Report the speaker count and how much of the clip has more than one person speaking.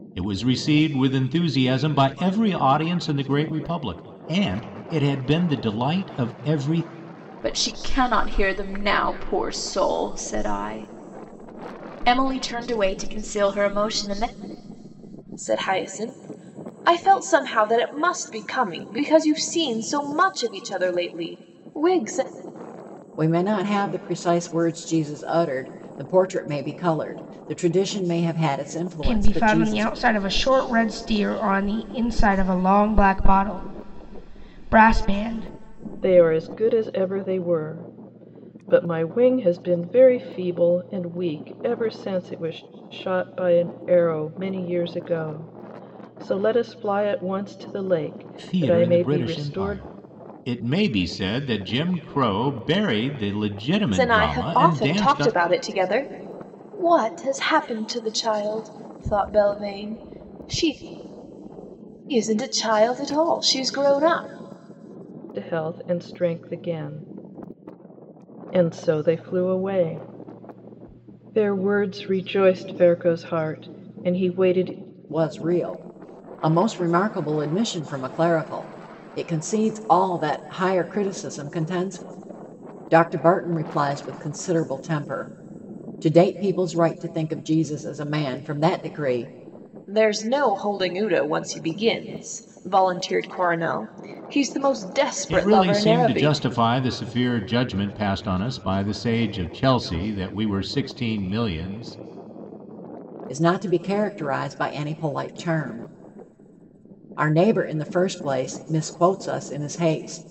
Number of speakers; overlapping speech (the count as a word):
six, about 4%